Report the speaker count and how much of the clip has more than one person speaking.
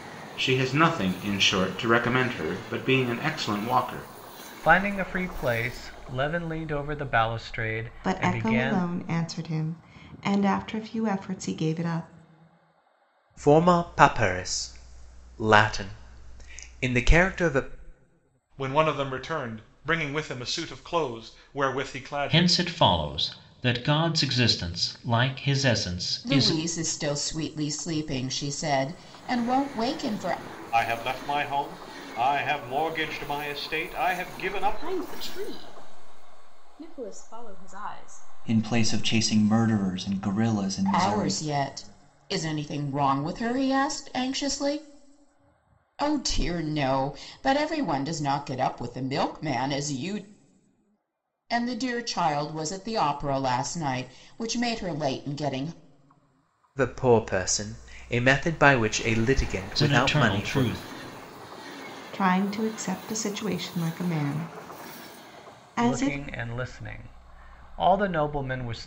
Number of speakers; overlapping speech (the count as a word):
ten, about 6%